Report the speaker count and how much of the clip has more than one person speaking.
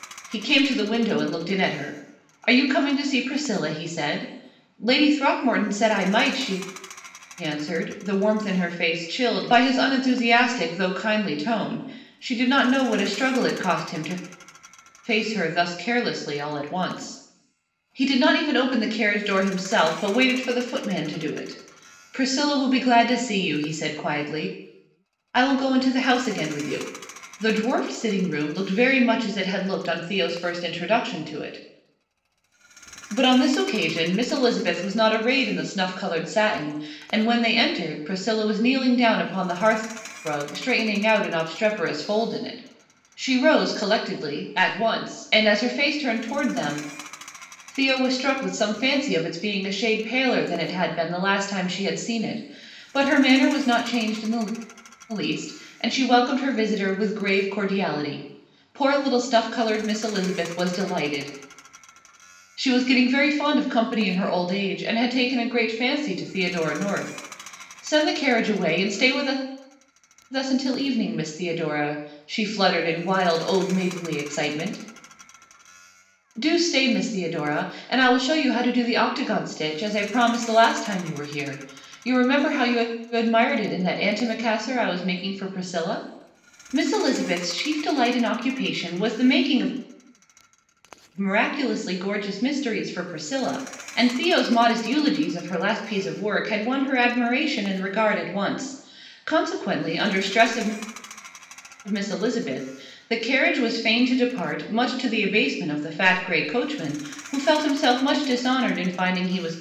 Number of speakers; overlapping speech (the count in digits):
1, no overlap